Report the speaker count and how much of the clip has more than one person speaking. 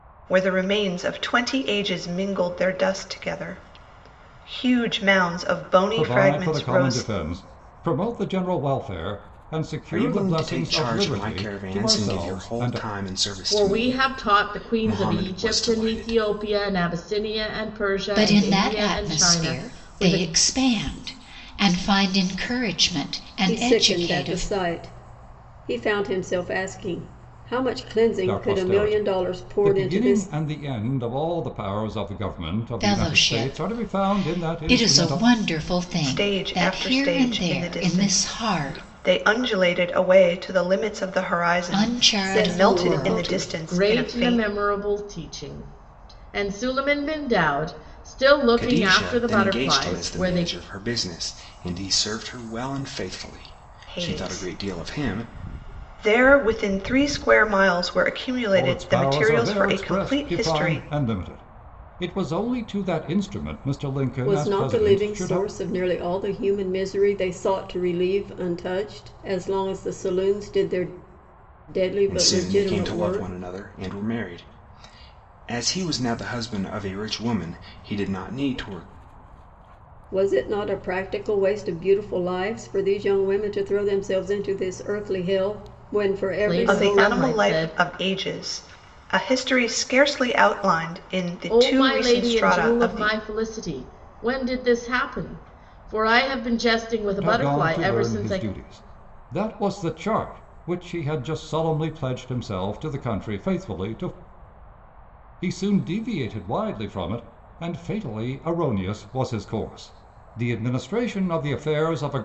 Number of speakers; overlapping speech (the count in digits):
6, about 30%